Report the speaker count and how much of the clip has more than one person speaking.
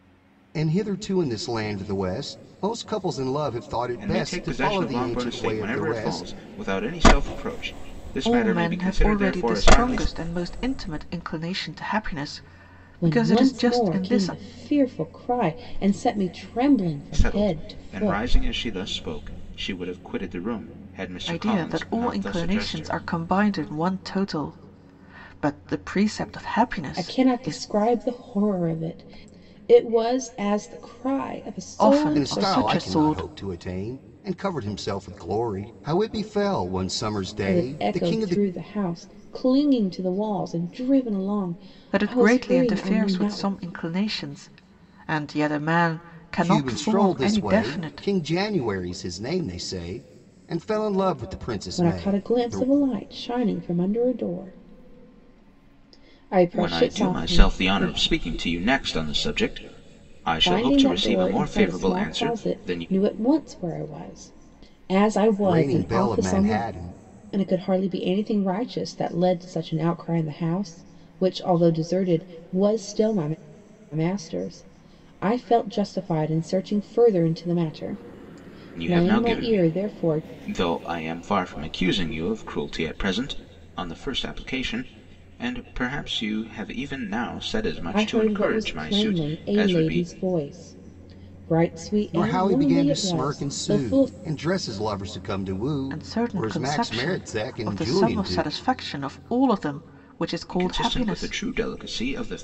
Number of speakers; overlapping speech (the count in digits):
4, about 30%